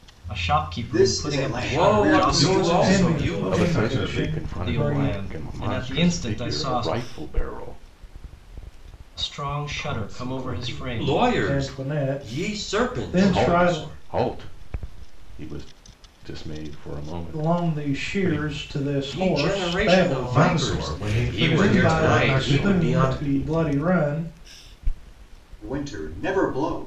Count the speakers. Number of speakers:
6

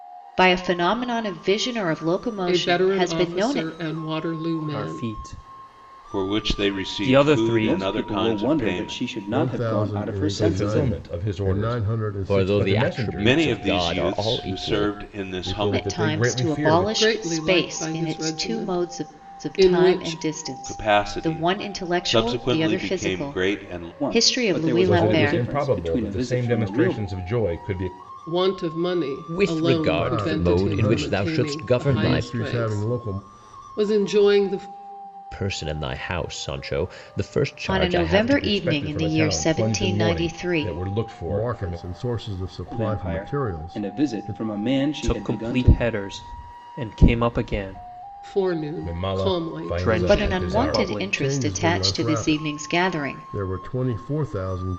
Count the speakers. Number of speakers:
8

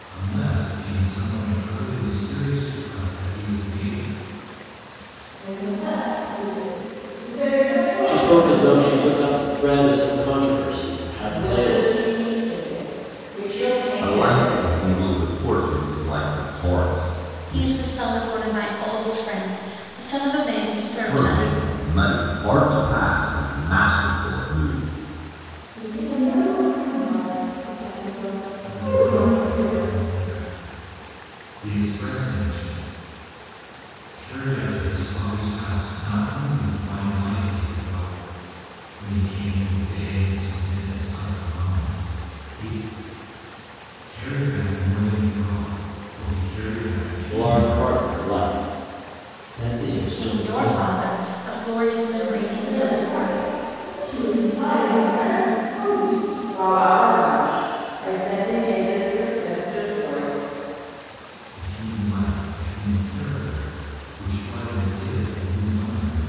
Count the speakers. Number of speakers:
6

